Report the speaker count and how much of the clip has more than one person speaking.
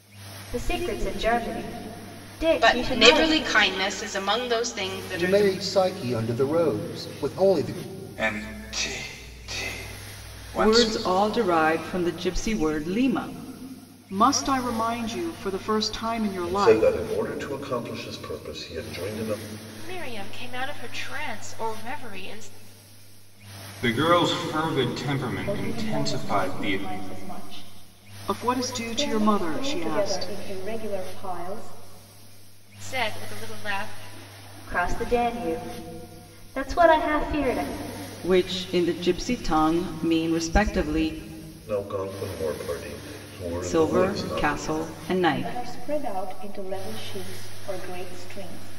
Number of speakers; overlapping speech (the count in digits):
10, about 13%